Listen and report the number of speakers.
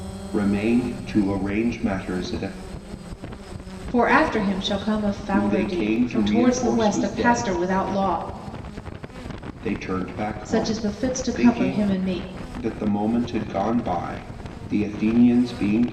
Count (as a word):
two